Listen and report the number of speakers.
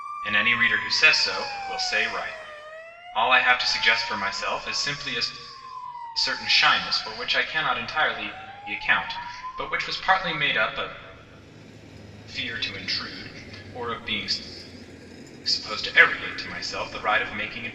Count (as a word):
one